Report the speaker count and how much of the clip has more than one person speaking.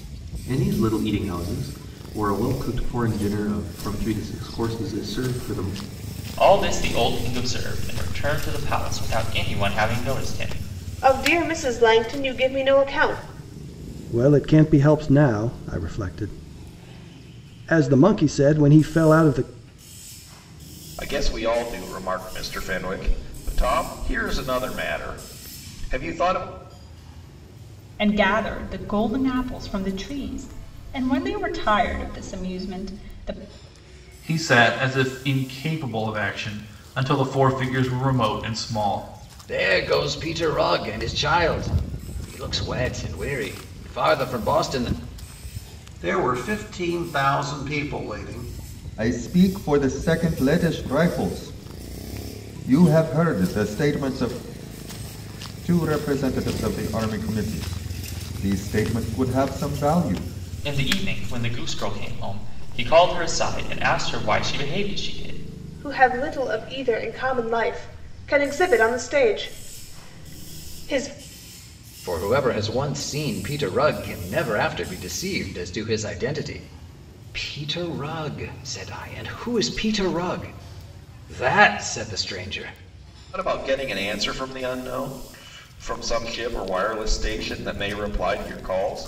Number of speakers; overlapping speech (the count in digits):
10, no overlap